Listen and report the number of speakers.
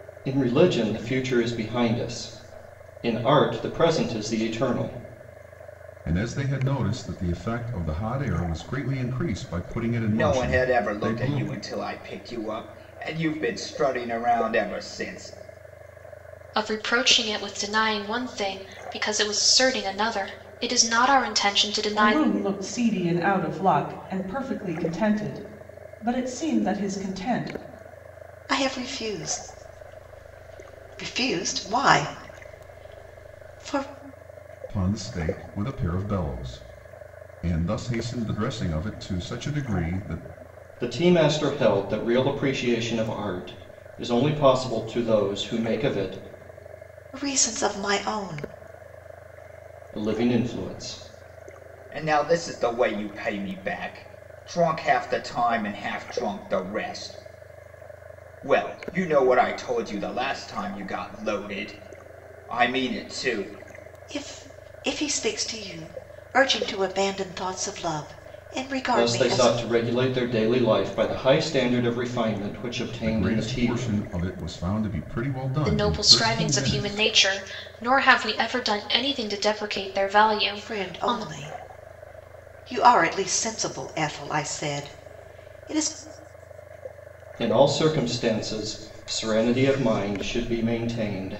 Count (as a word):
six